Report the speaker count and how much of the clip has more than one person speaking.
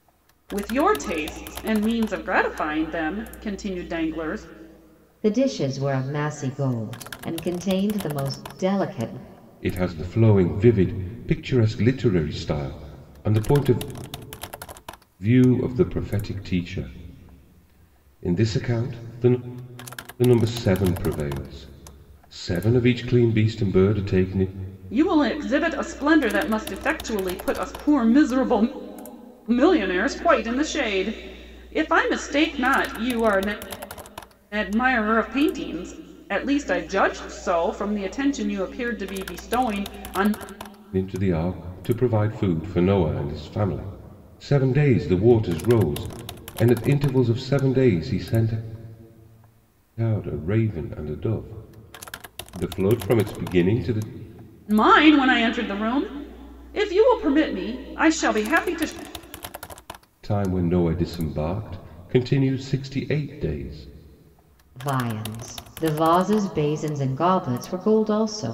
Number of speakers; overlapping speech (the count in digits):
3, no overlap